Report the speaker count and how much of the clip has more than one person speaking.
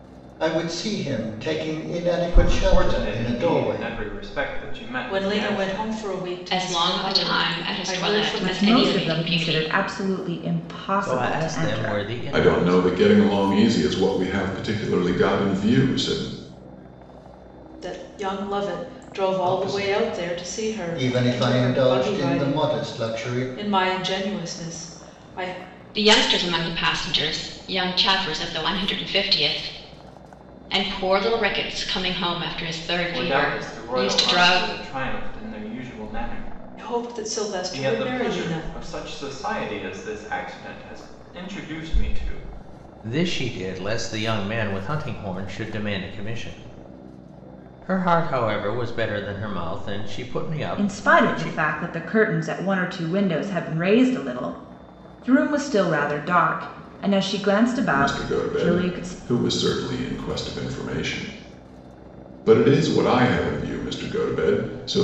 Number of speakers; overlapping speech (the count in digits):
7, about 25%